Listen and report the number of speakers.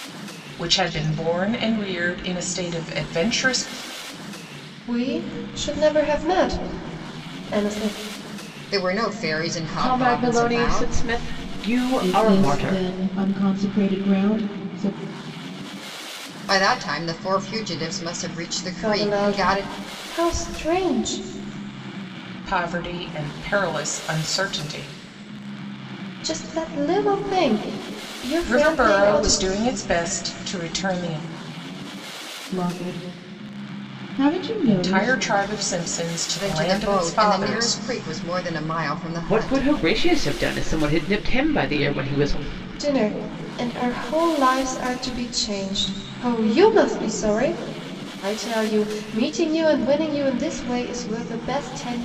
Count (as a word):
five